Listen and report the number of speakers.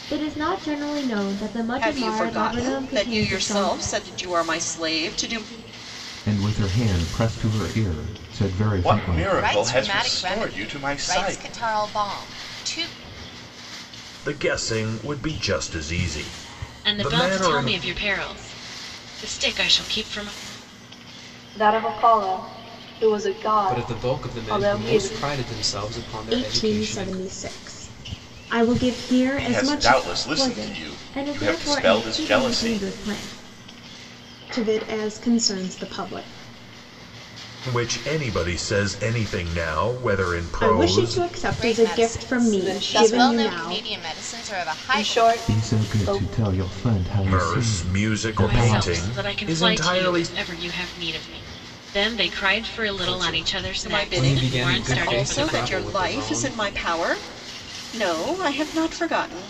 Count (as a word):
ten